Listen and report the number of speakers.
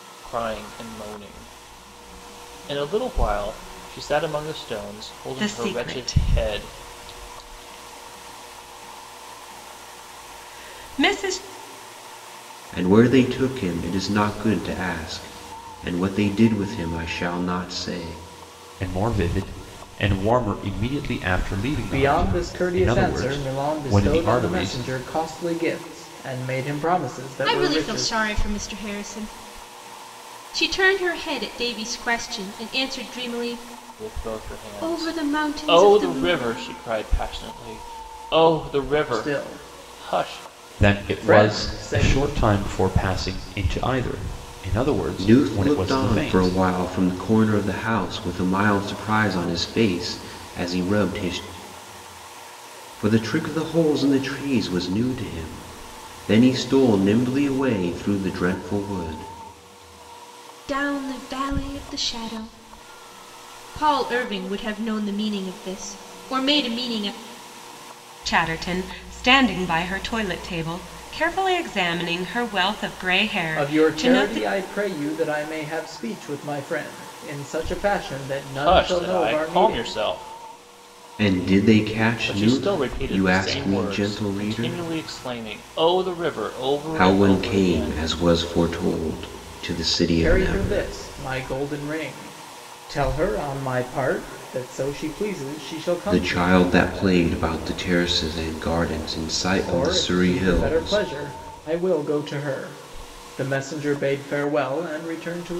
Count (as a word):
six